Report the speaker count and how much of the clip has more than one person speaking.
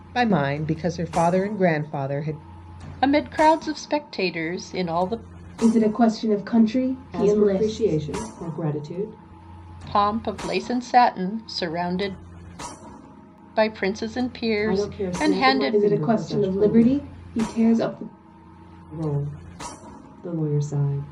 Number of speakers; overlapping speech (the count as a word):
four, about 15%